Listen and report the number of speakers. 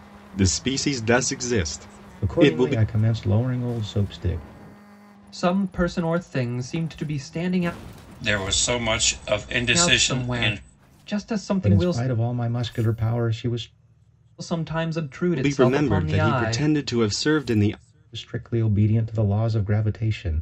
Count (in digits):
4